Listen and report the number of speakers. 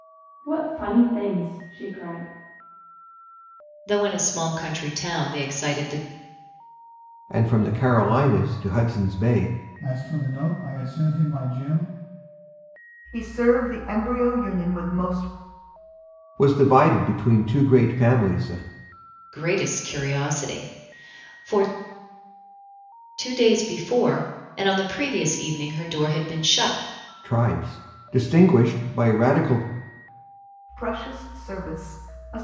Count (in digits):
5